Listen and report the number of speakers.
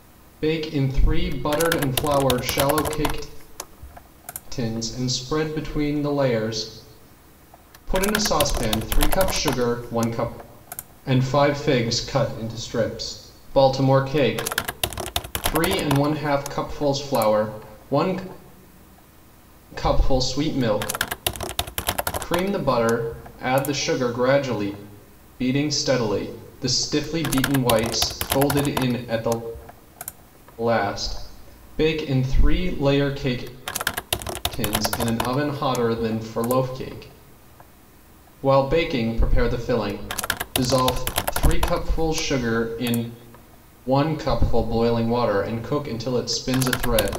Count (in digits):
1